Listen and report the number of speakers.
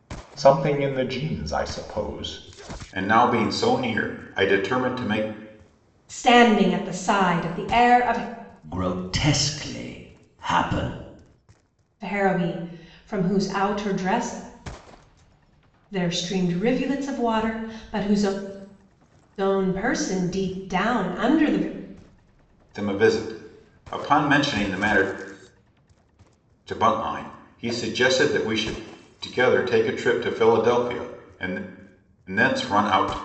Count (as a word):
four